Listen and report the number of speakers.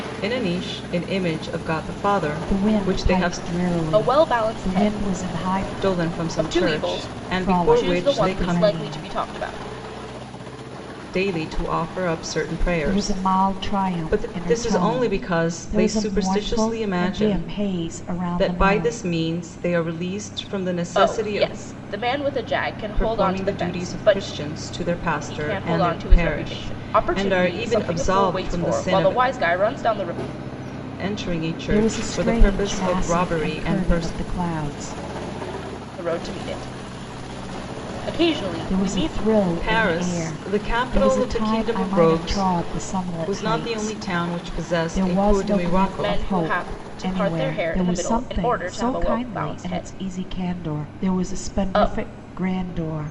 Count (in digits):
3